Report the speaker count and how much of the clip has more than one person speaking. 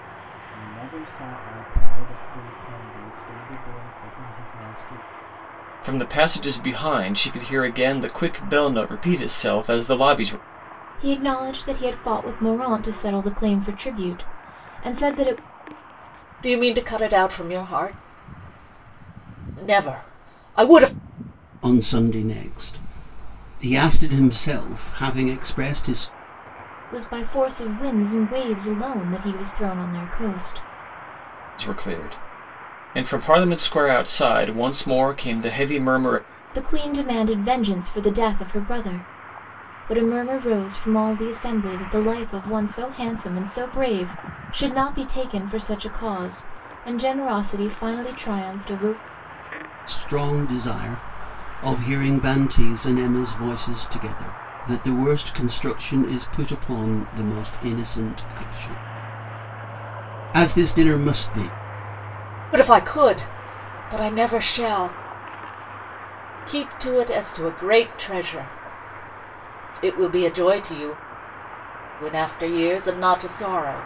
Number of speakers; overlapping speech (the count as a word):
five, no overlap